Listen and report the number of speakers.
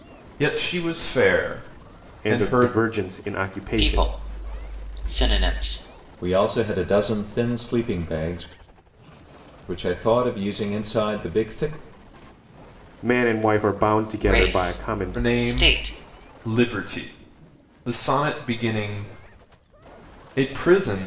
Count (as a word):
four